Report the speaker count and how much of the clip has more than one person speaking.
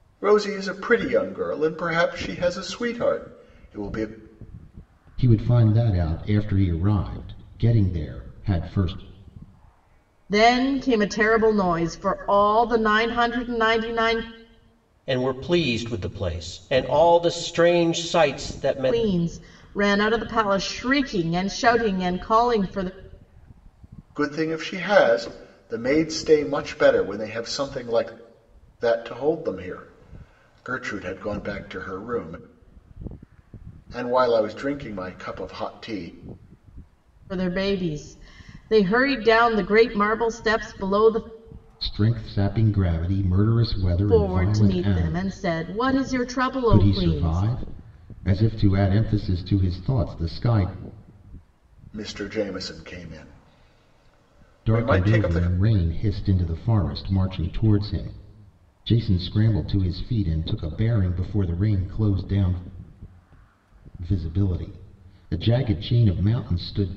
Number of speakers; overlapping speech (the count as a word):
four, about 5%